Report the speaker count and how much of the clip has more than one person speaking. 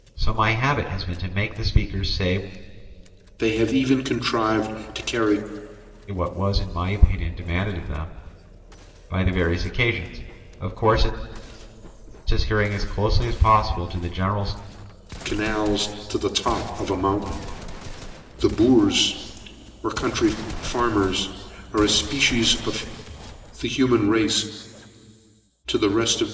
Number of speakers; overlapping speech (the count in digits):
2, no overlap